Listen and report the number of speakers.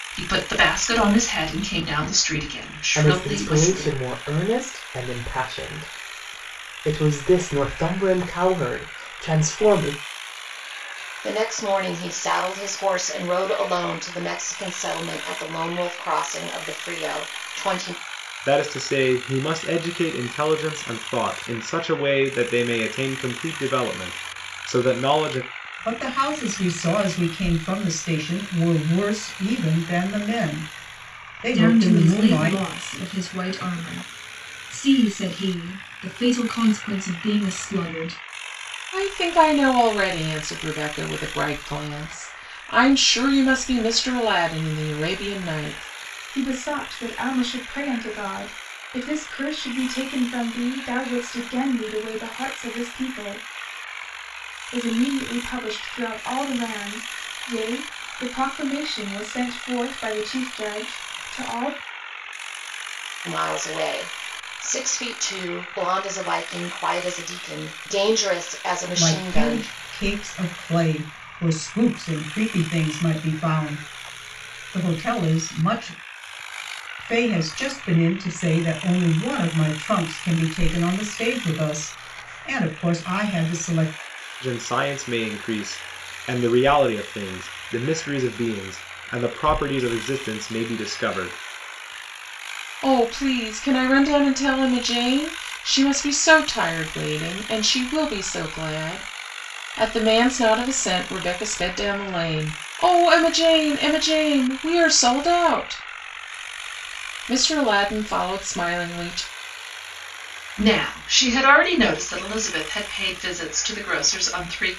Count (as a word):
eight